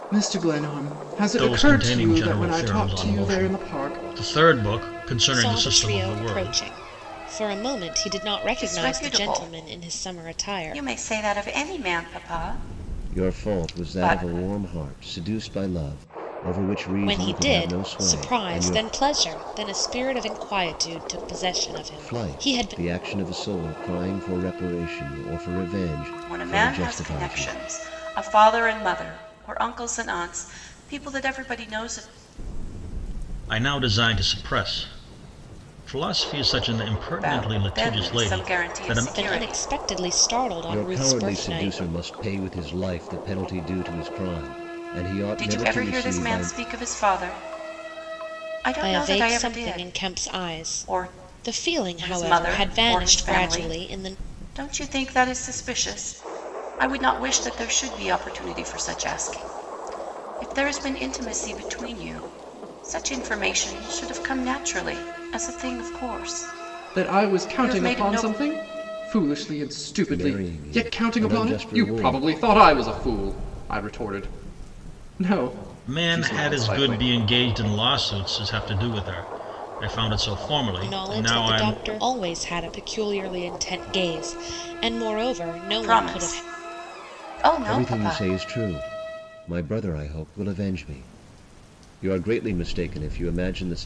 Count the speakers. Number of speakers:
5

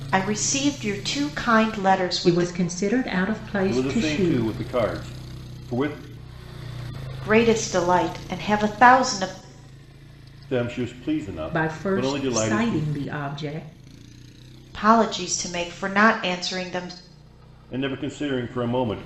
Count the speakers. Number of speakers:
3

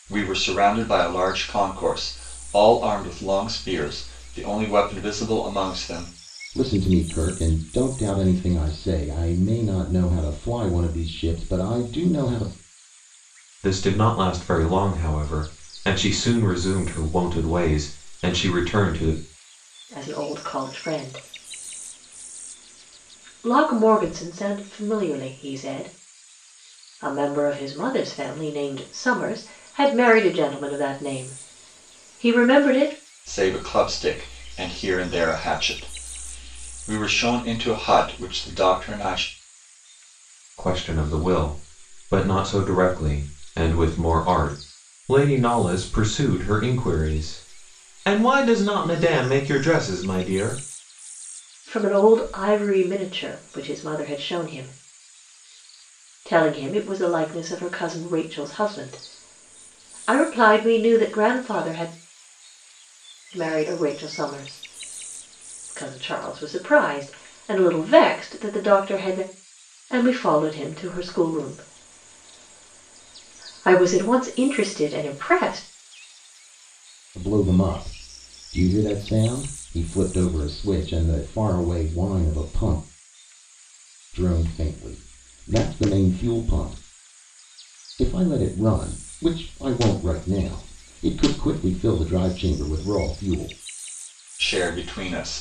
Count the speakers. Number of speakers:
4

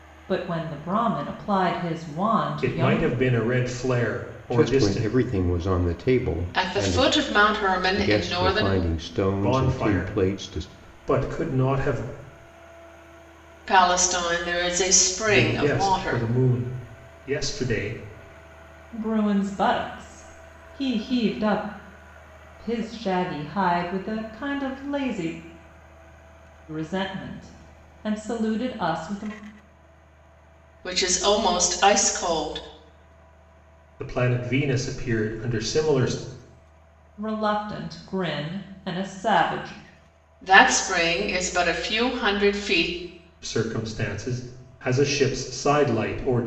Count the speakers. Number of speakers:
4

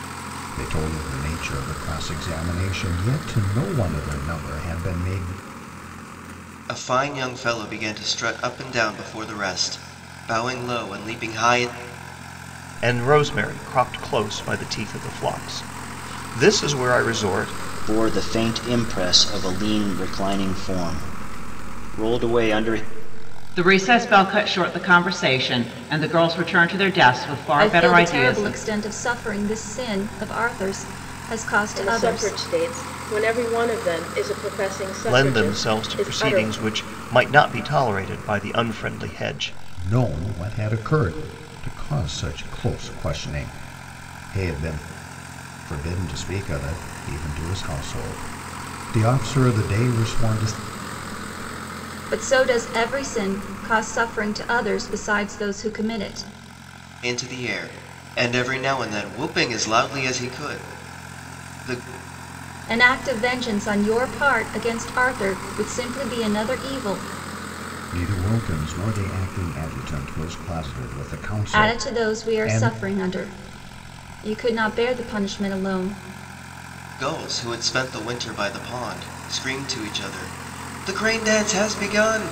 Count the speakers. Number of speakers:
7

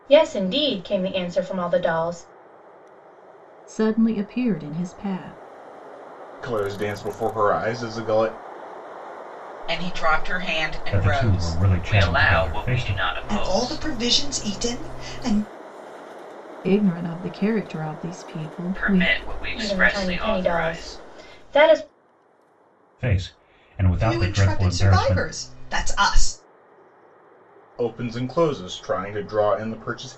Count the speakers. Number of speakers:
7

